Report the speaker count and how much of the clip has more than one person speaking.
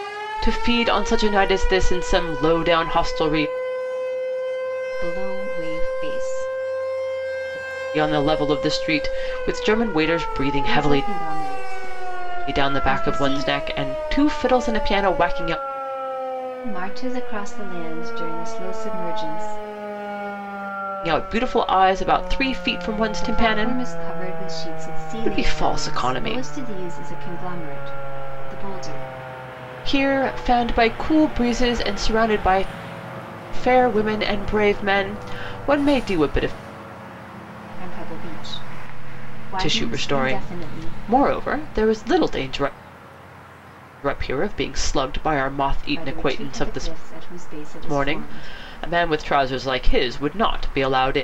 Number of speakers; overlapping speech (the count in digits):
2, about 13%